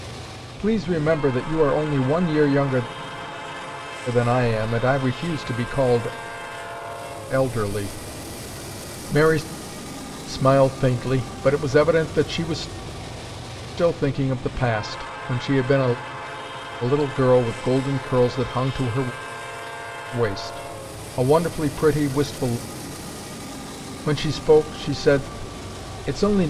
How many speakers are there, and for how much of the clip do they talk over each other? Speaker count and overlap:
1, no overlap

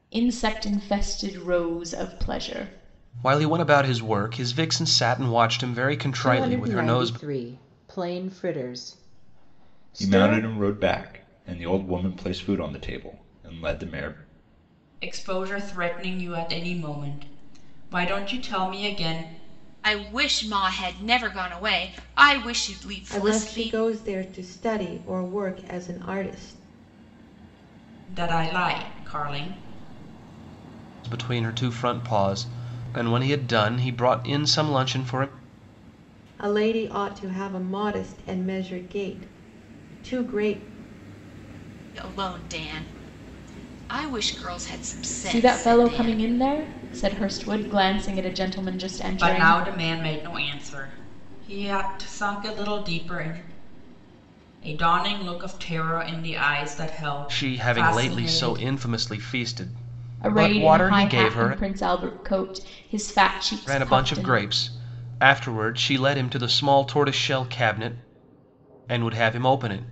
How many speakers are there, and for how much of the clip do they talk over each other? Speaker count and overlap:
7, about 10%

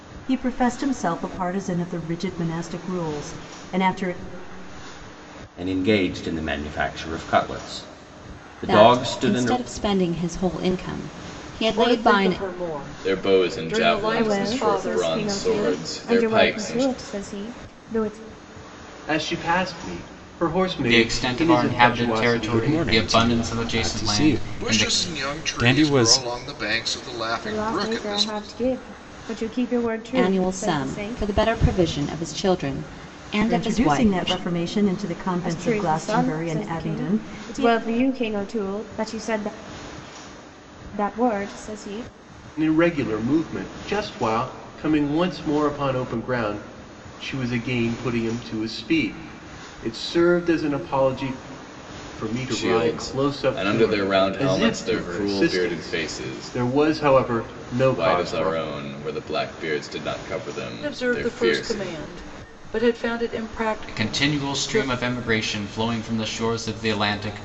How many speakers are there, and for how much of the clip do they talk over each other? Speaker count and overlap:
10, about 34%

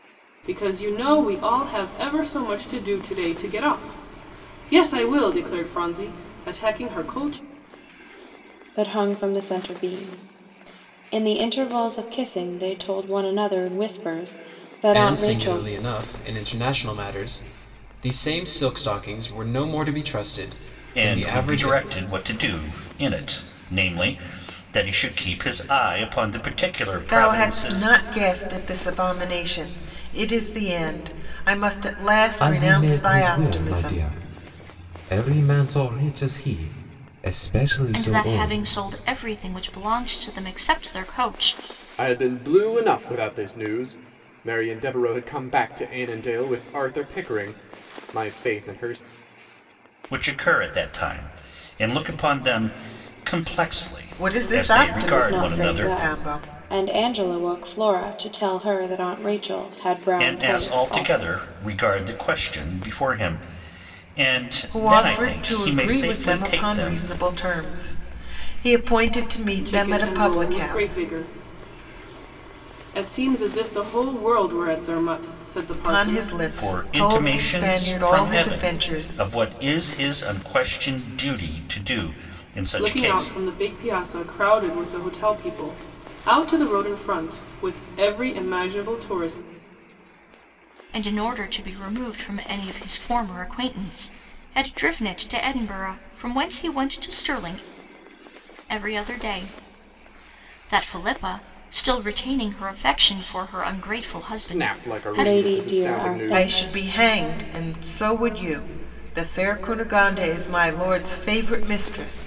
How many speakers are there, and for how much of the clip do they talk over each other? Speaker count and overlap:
8, about 16%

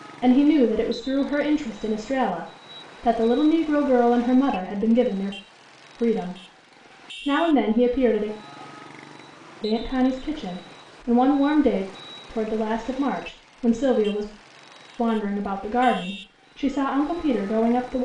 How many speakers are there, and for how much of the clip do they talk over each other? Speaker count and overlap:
1, no overlap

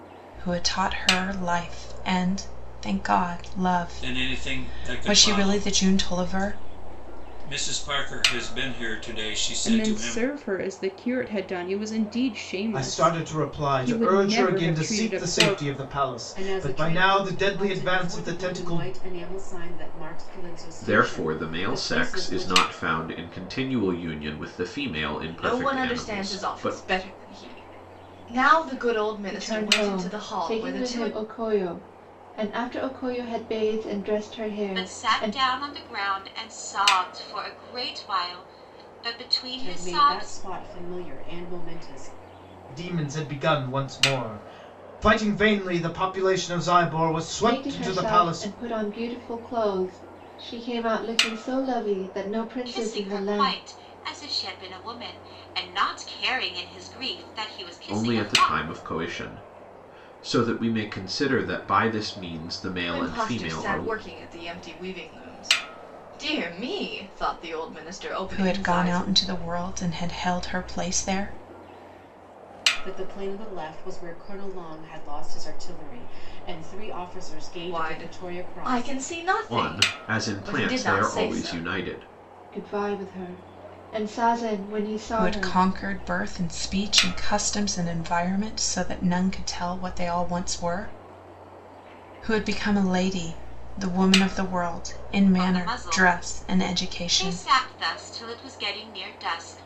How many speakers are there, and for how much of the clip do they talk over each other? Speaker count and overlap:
9, about 27%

